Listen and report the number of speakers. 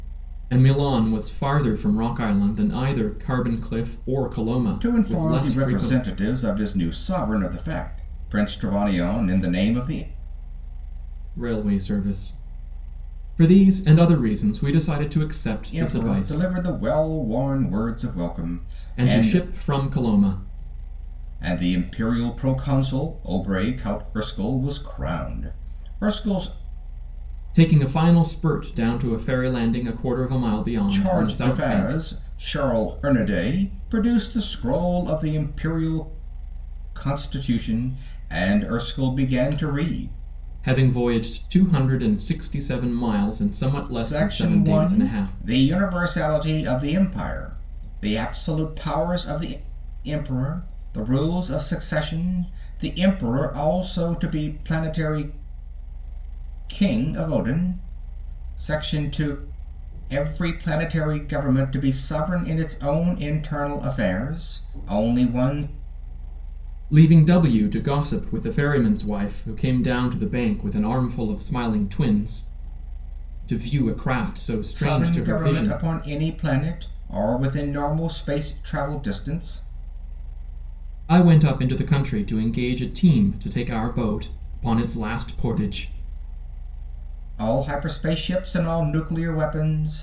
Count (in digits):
2